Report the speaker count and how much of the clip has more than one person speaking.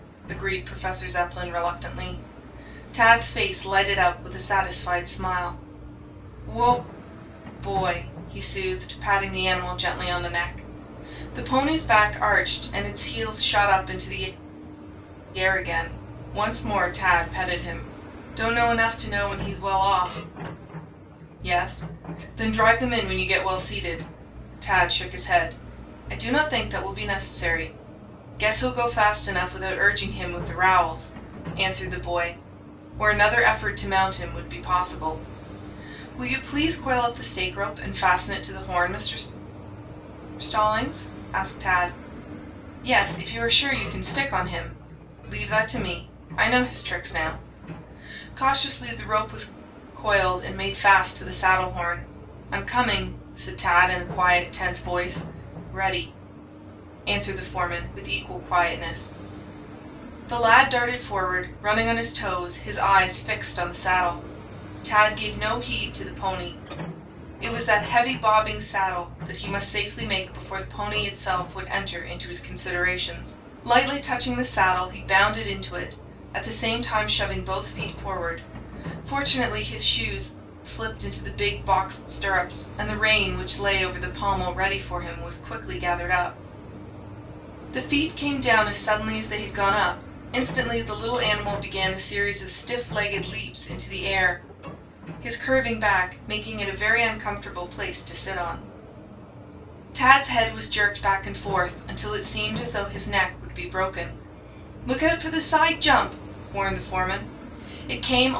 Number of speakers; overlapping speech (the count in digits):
1, no overlap